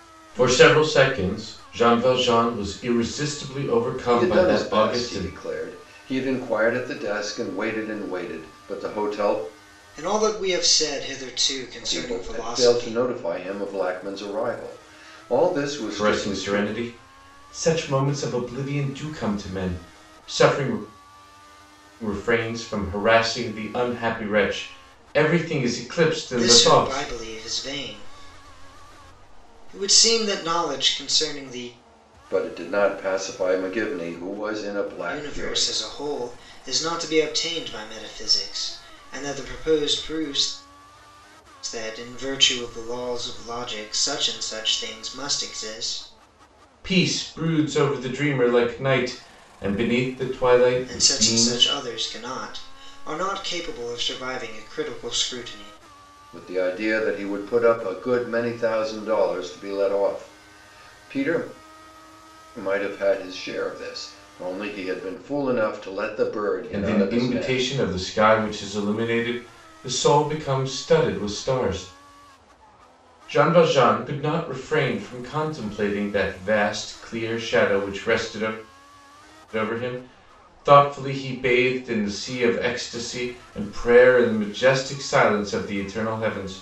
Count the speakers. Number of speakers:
three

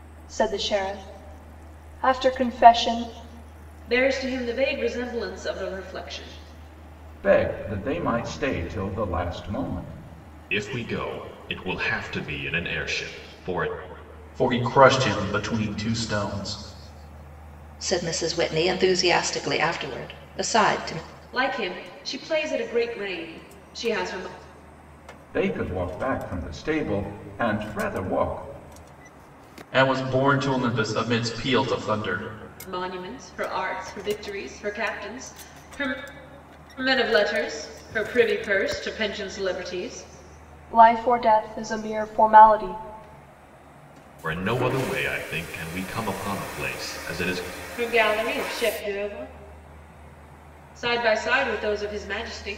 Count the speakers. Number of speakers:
six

